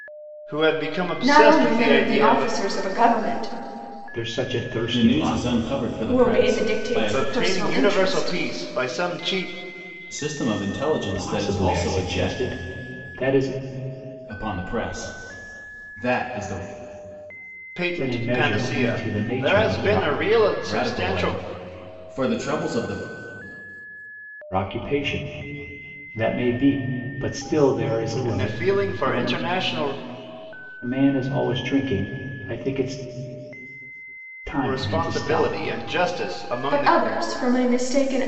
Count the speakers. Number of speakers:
four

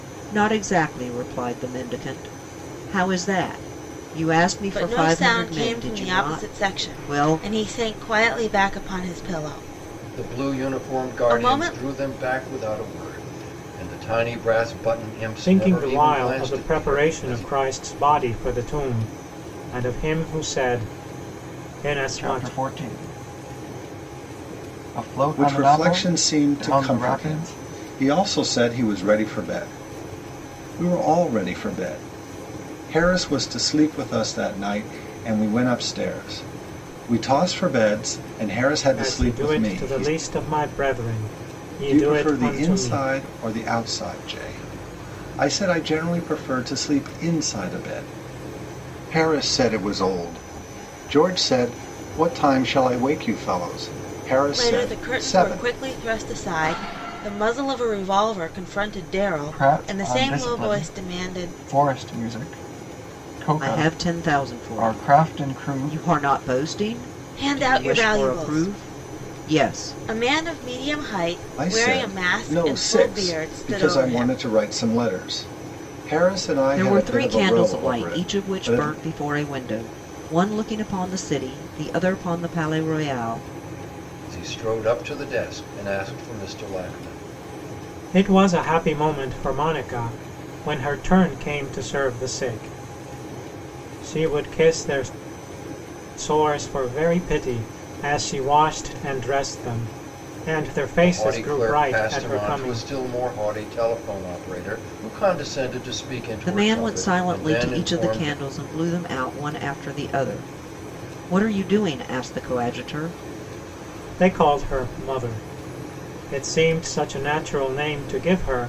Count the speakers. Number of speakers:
six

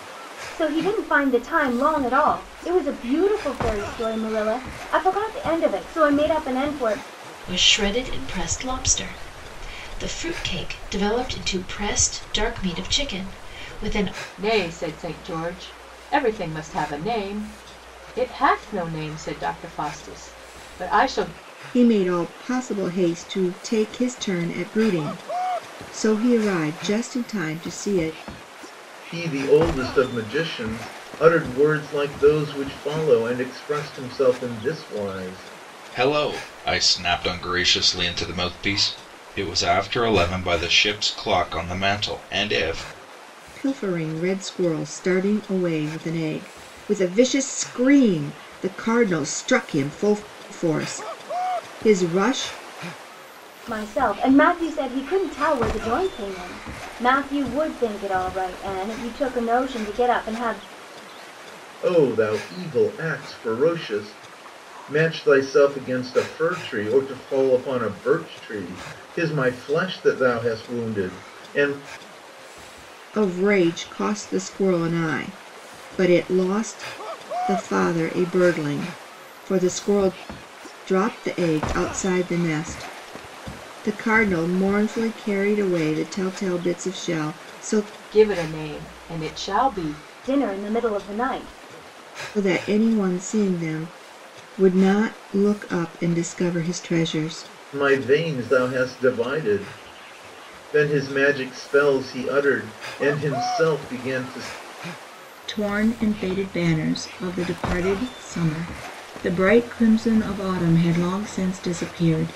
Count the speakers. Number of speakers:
six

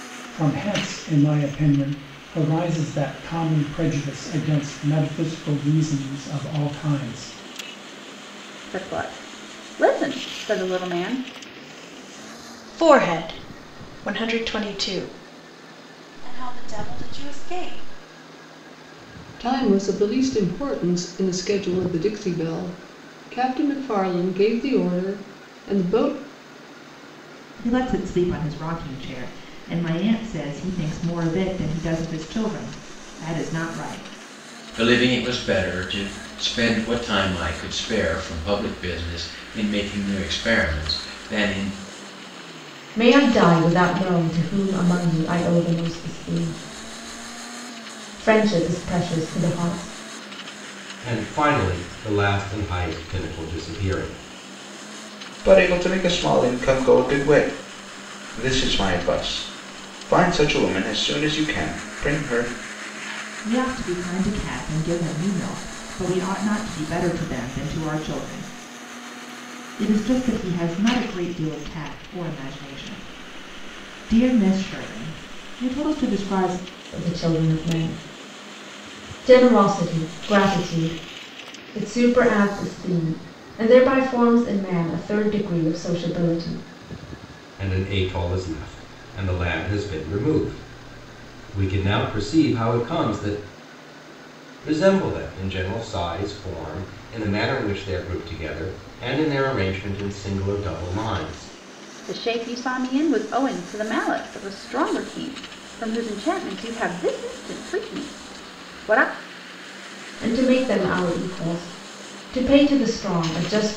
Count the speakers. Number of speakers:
ten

